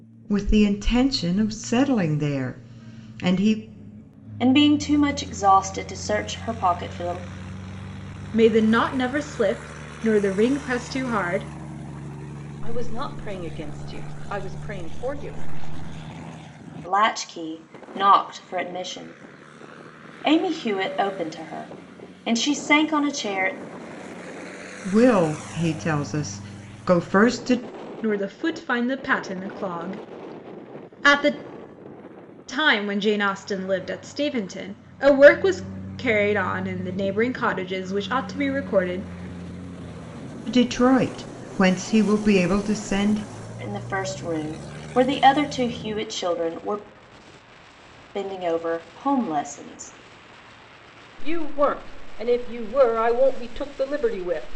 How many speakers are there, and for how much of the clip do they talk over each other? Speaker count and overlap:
4, no overlap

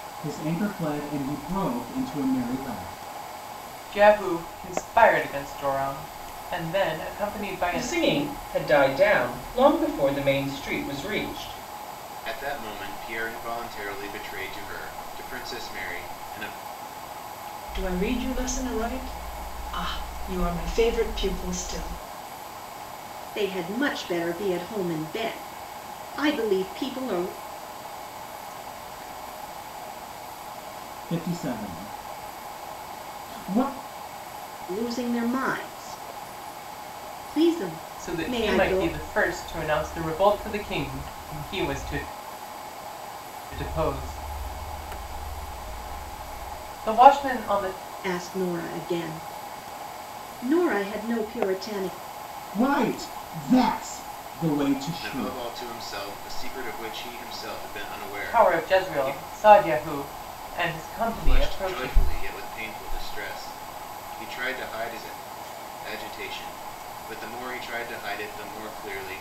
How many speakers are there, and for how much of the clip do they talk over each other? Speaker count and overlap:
6, about 5%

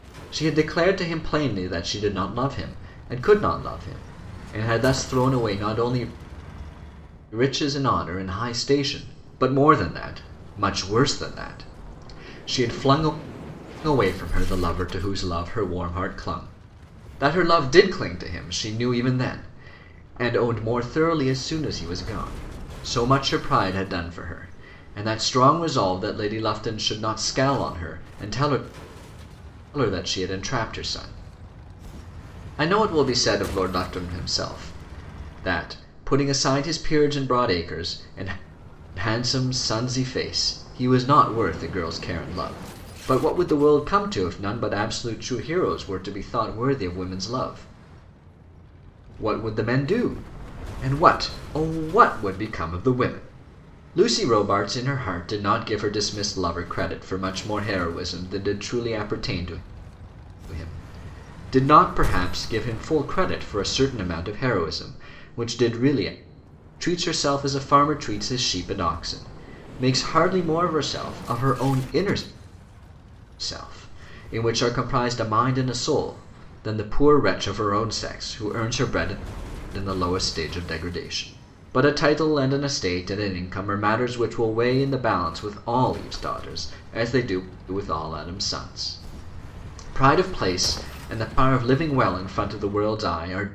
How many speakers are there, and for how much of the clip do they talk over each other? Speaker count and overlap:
1, no overlap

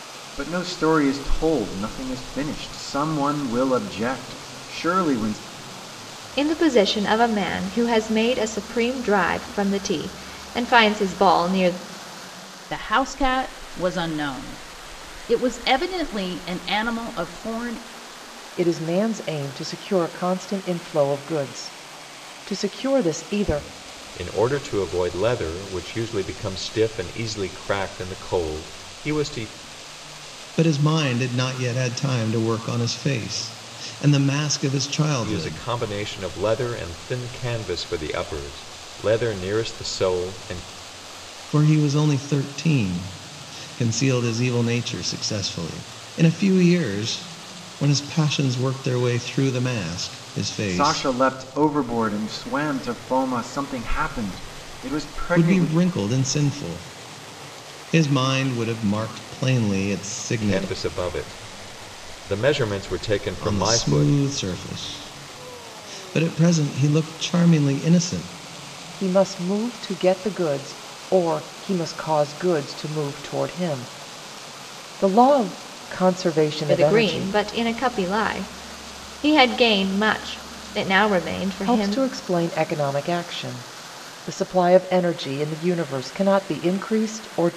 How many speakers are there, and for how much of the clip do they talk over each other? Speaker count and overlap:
6, about 4%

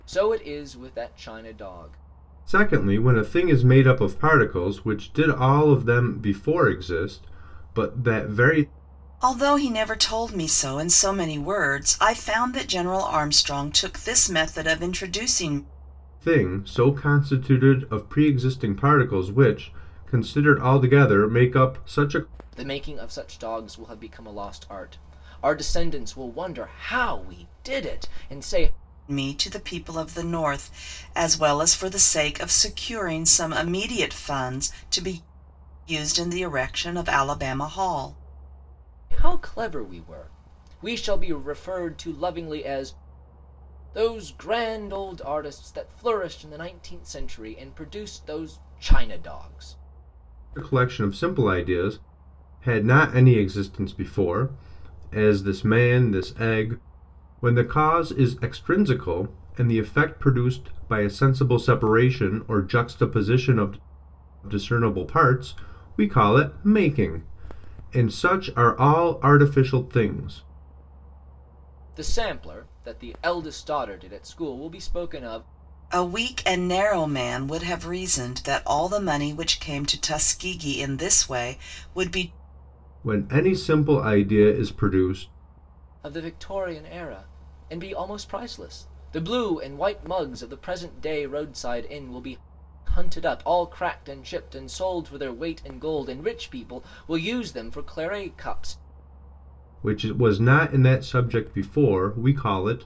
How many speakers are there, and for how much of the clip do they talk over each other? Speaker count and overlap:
3, no overlap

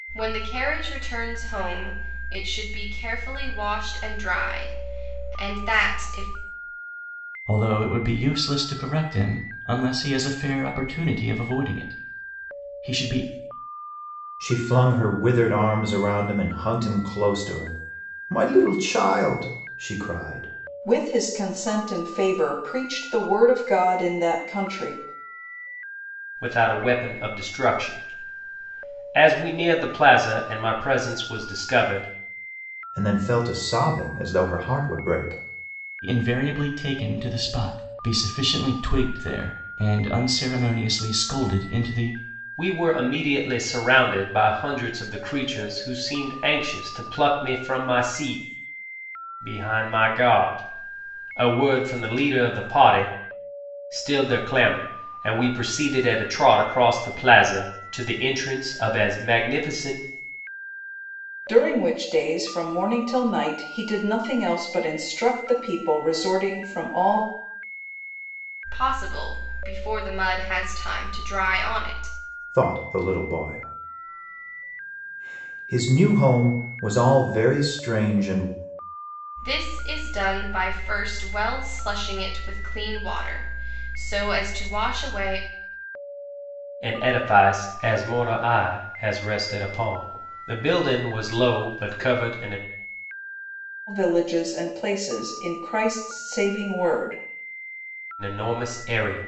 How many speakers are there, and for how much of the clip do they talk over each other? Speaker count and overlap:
5, no overlap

